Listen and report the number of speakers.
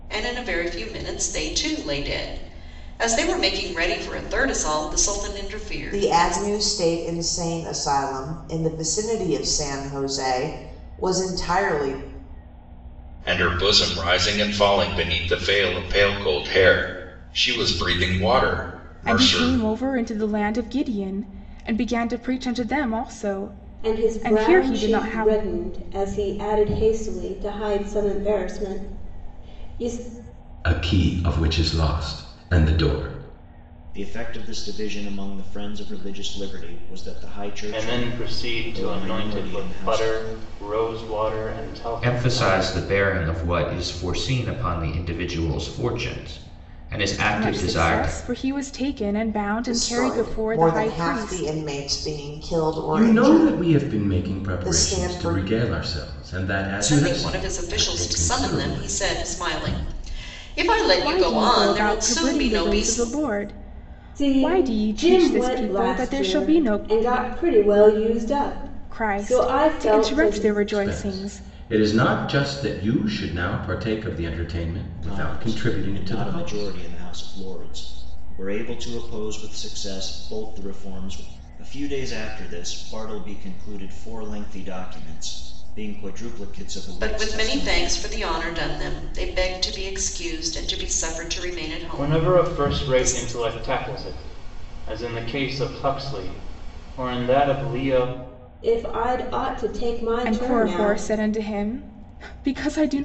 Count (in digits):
9